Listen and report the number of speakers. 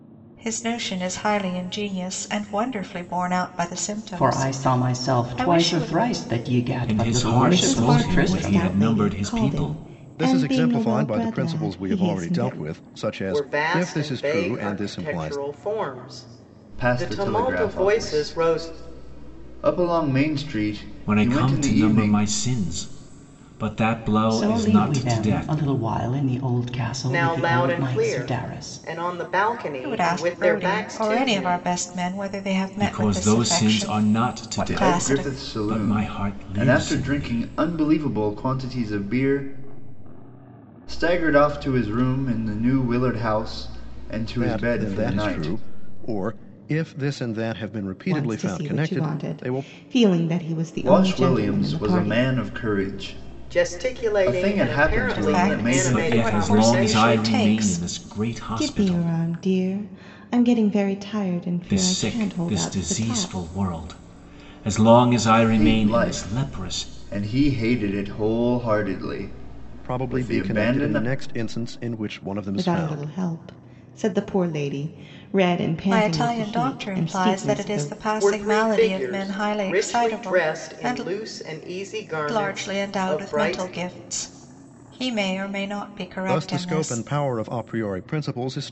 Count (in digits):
7